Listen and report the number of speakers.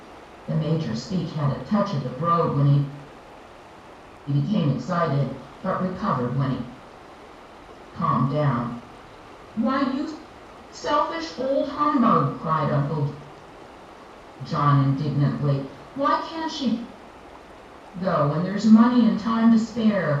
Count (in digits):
1